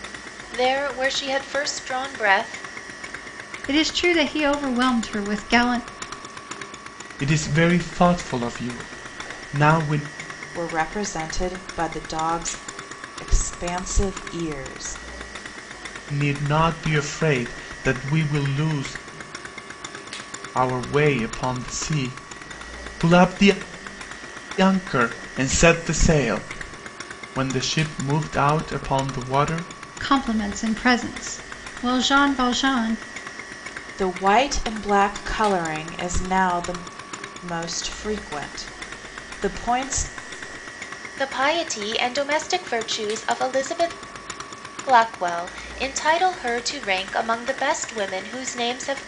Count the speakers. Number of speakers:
4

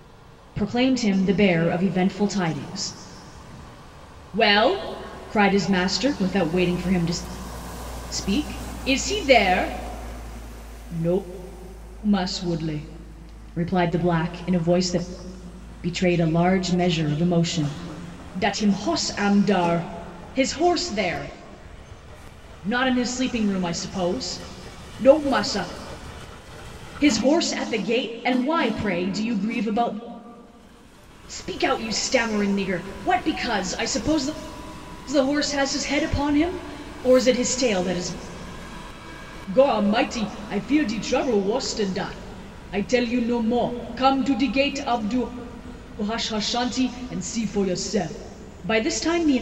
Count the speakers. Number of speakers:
1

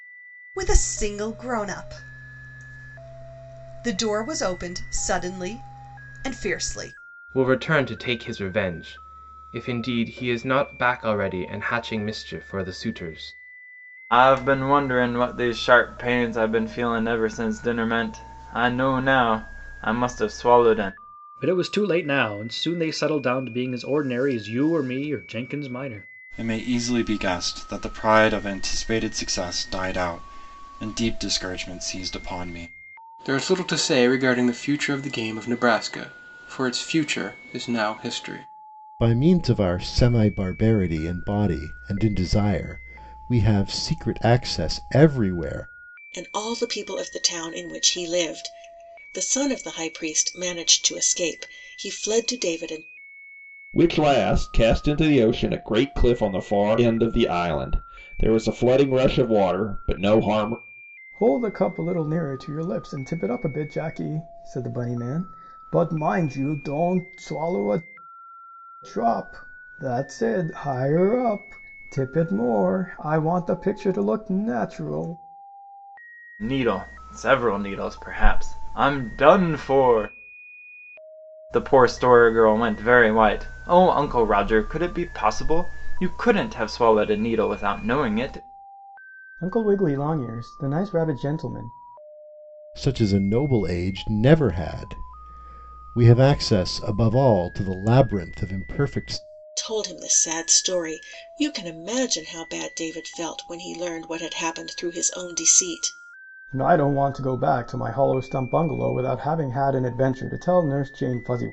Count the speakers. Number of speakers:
10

